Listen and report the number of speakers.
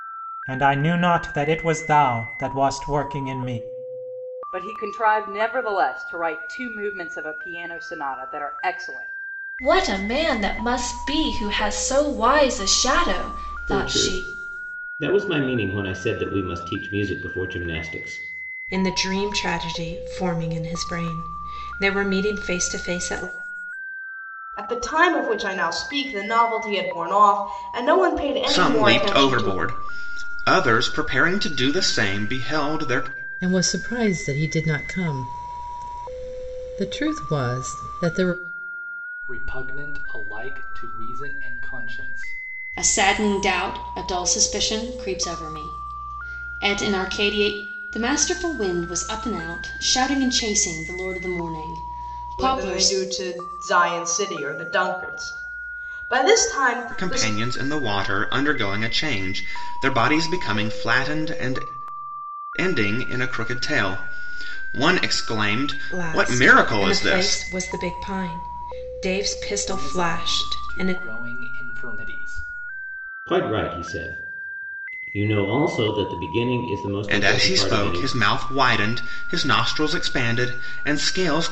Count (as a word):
ten